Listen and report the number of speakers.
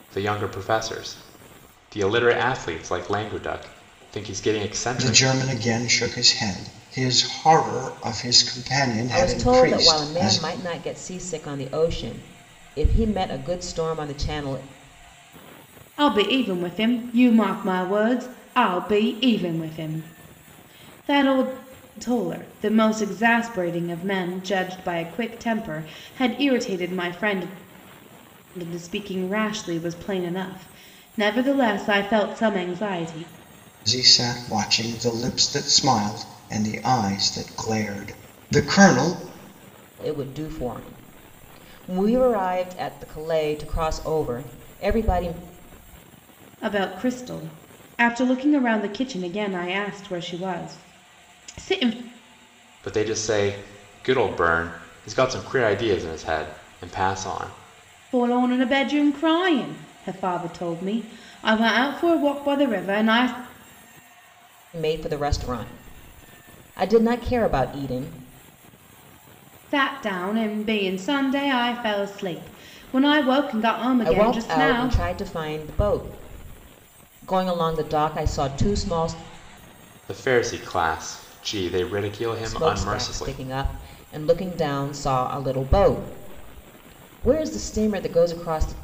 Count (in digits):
4